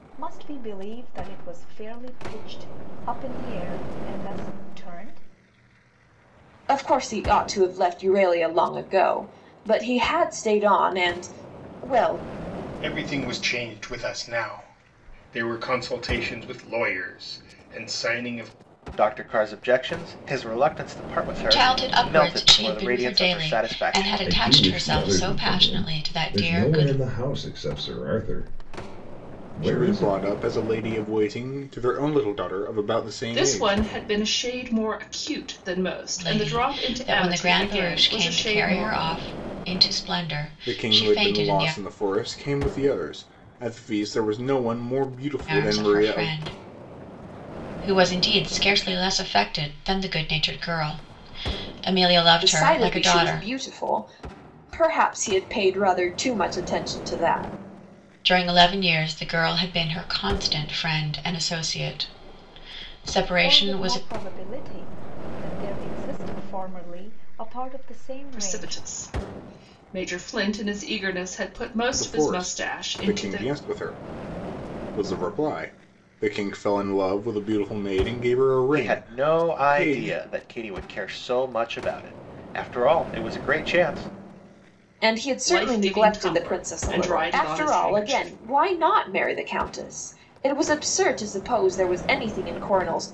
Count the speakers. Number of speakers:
8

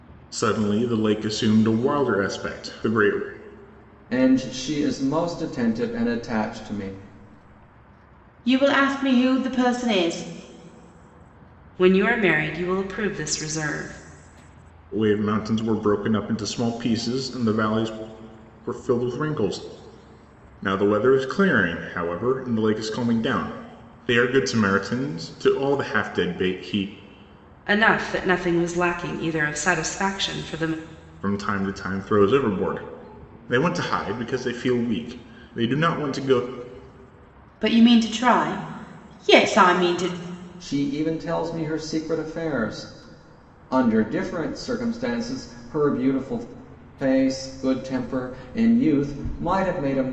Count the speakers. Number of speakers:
4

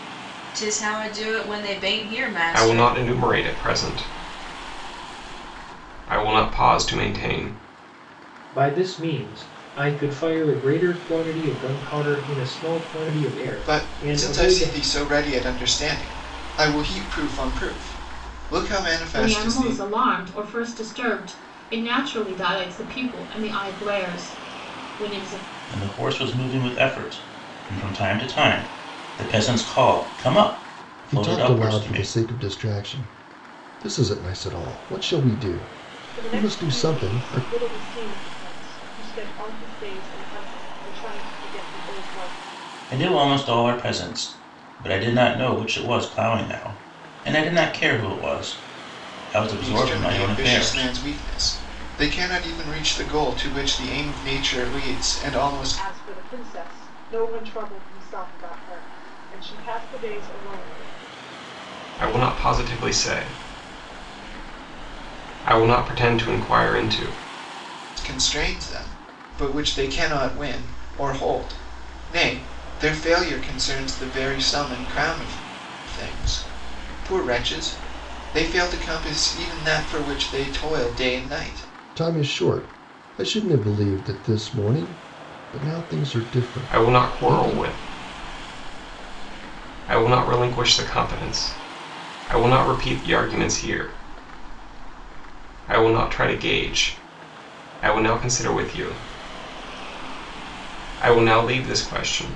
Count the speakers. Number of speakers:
8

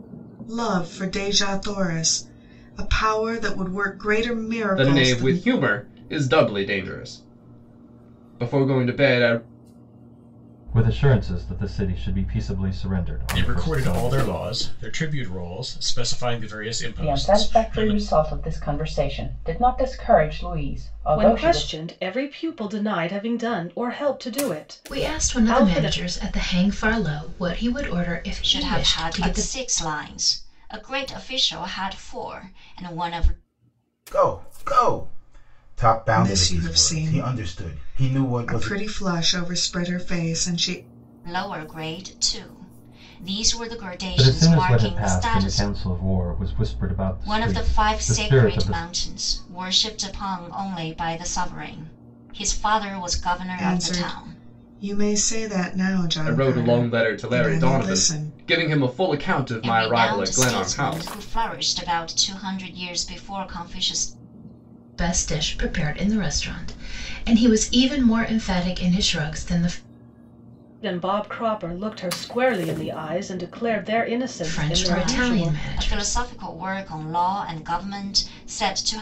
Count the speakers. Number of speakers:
9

